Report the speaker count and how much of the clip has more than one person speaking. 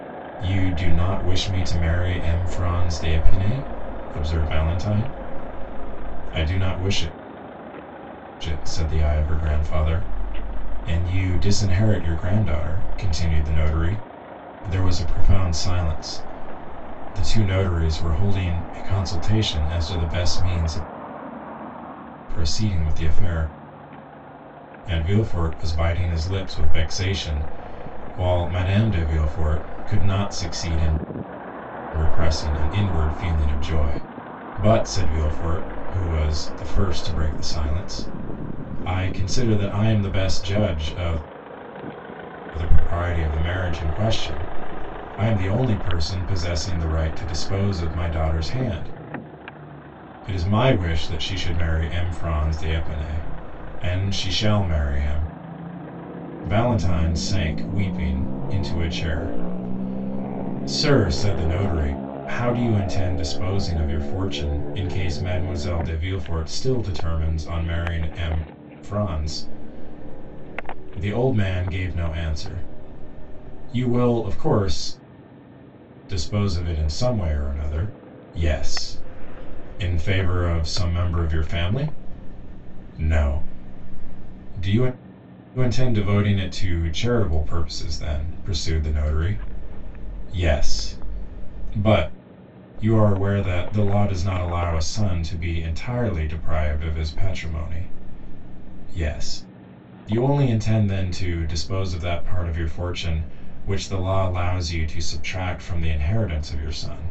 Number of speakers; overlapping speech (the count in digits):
1, no overlap